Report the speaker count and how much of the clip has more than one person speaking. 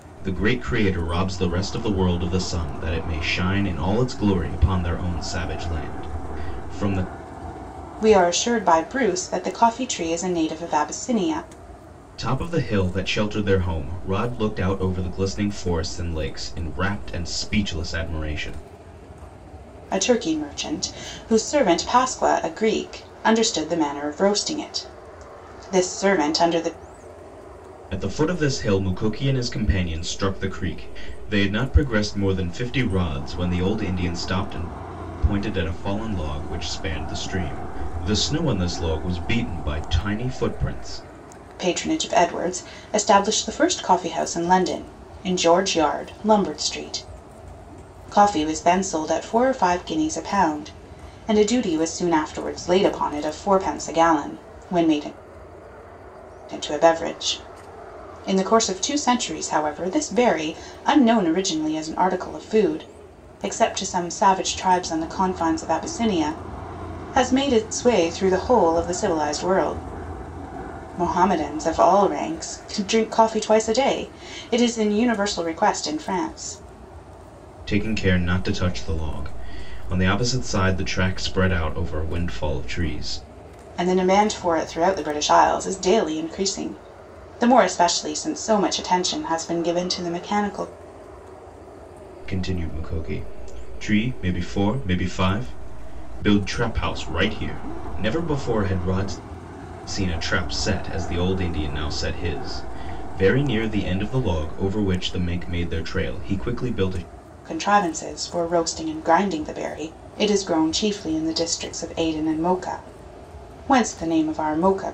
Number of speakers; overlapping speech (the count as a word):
two, no overlap